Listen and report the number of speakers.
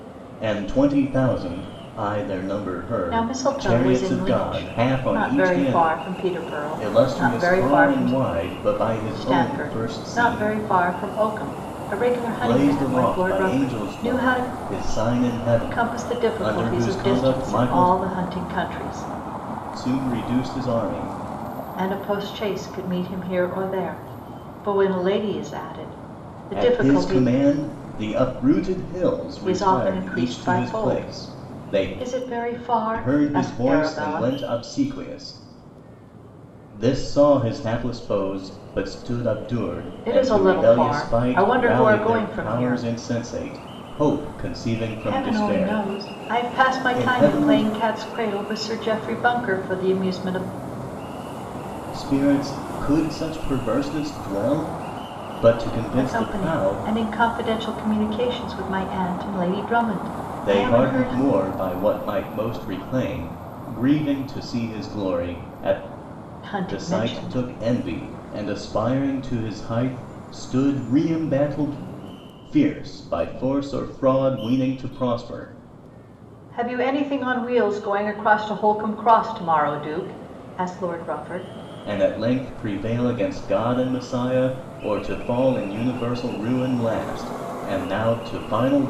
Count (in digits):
2